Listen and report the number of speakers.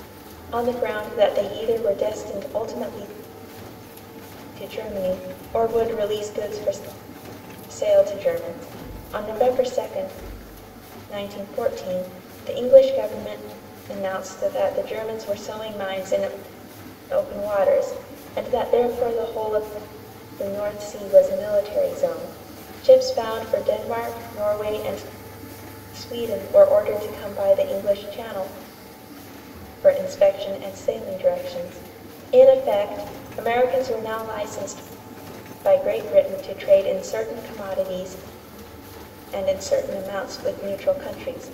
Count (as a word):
one